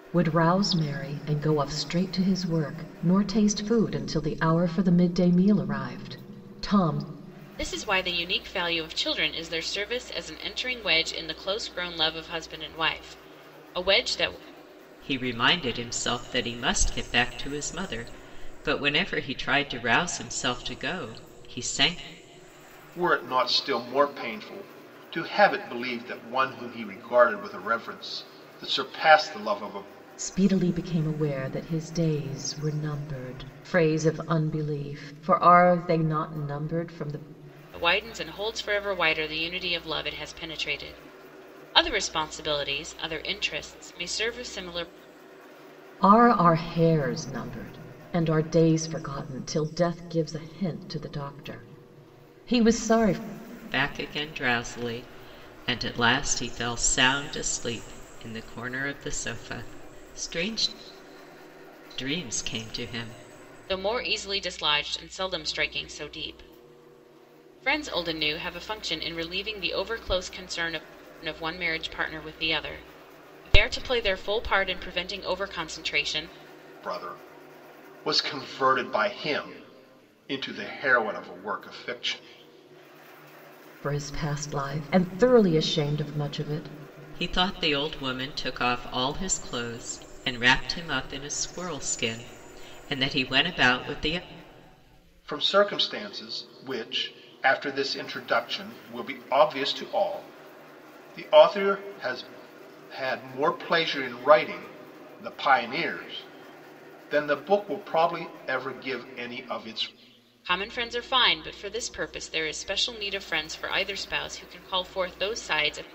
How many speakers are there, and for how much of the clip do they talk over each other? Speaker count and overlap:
four, no overlap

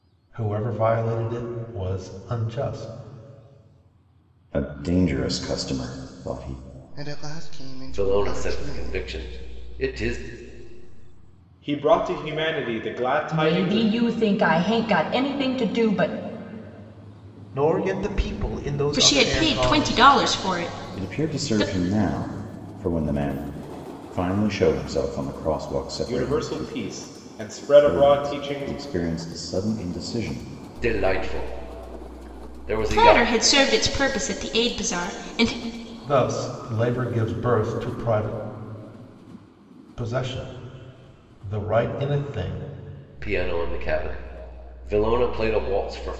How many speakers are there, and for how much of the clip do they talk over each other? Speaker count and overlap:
eight, about 13%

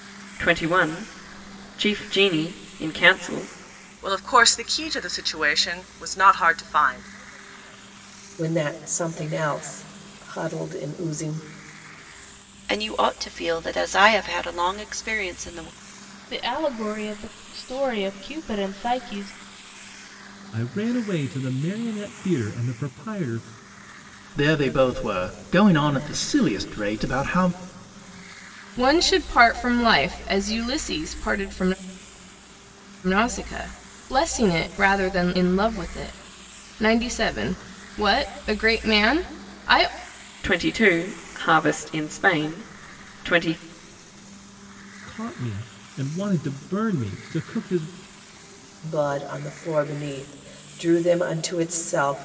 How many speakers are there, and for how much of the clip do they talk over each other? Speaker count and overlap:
eight, no overlap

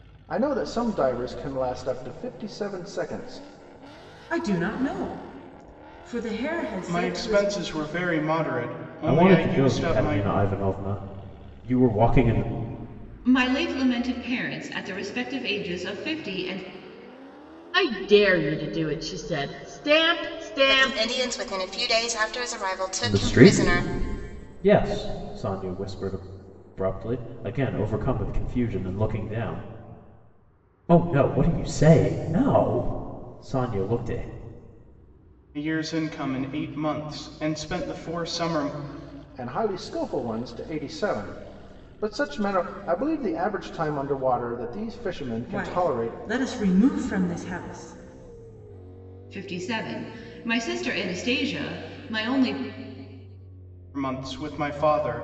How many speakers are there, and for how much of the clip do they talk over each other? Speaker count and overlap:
seven, about 7%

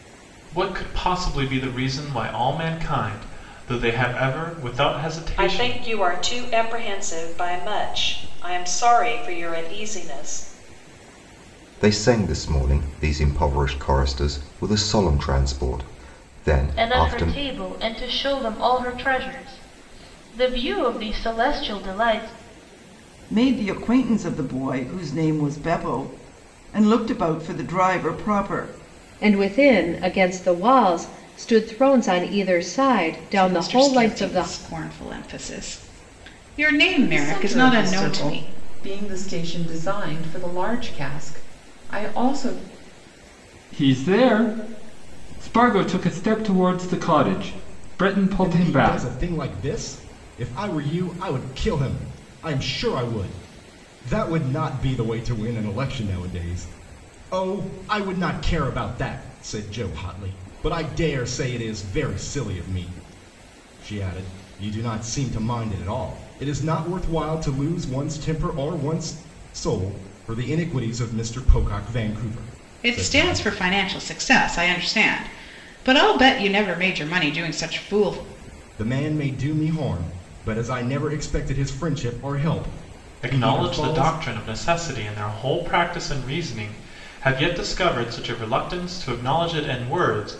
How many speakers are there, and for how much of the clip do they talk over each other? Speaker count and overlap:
ten, about 7%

